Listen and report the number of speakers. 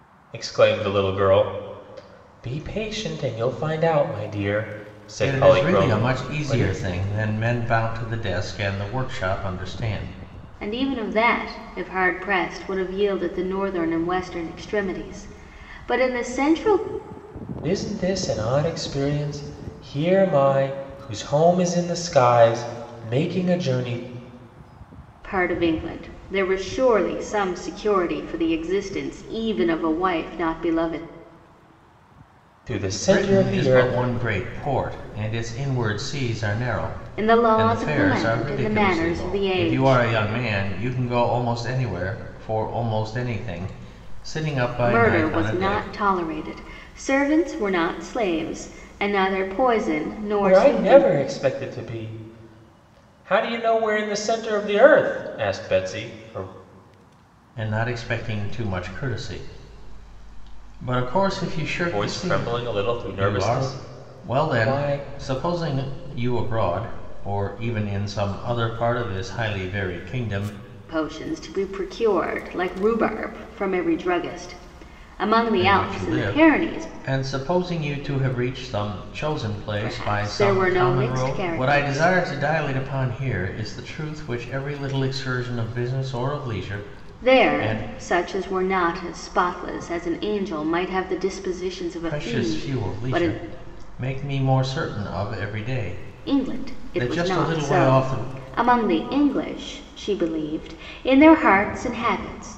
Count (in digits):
3